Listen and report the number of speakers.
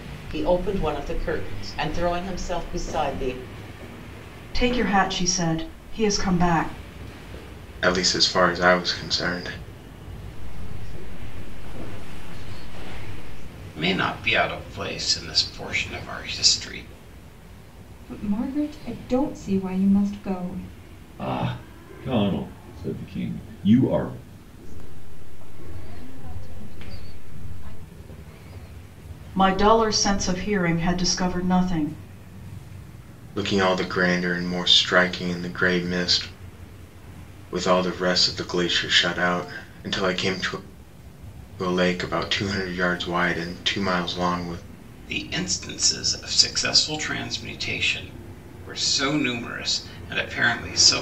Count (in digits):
7